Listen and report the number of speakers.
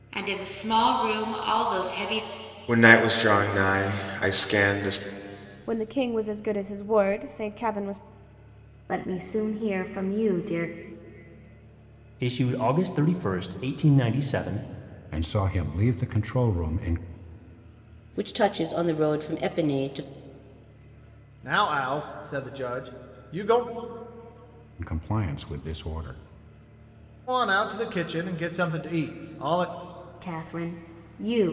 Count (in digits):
8